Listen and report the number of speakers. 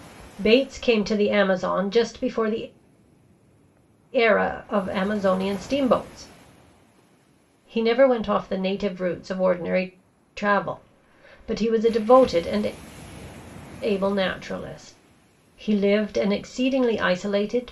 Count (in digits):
1